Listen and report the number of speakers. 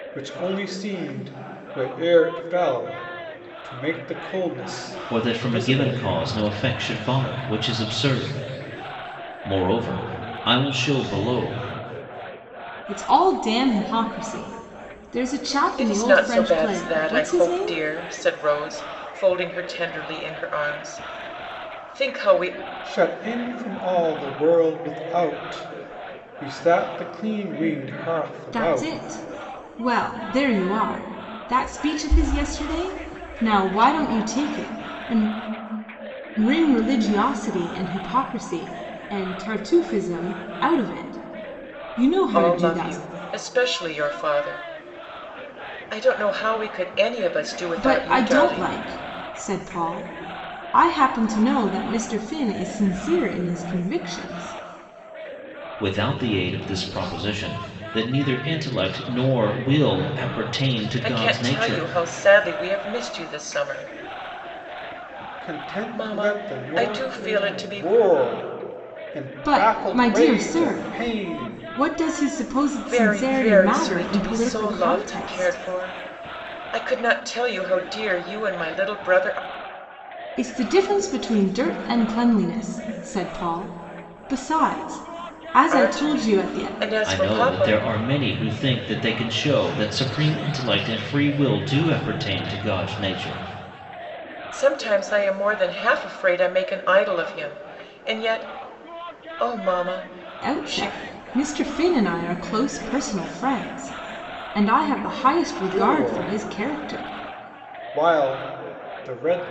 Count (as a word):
four